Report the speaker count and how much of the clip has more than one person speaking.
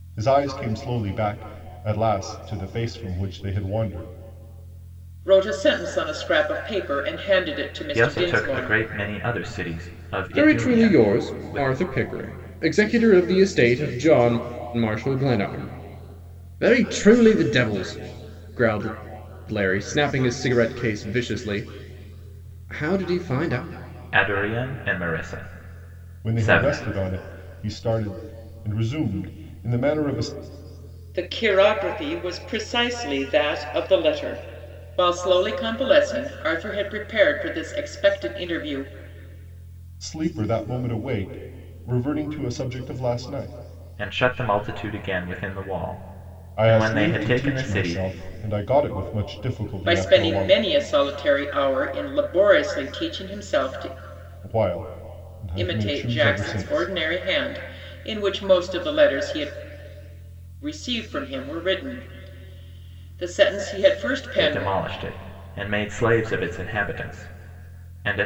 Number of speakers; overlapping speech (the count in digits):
4, about 10%